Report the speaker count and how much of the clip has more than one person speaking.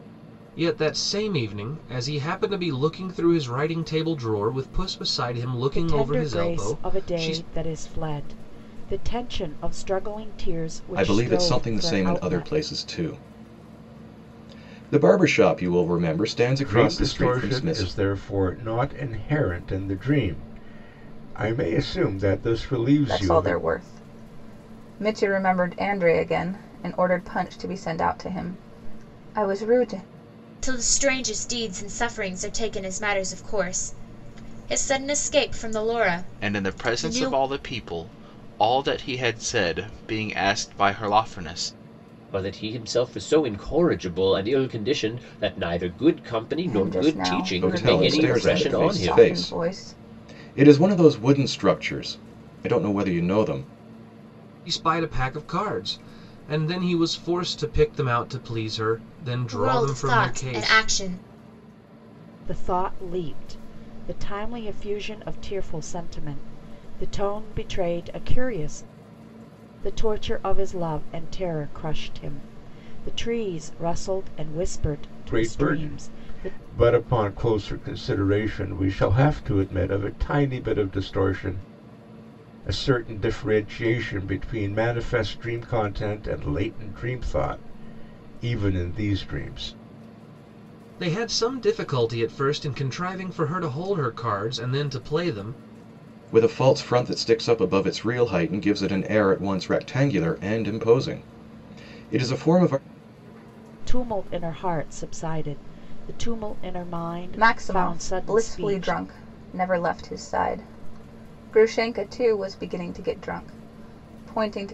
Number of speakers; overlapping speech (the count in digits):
8, about 12%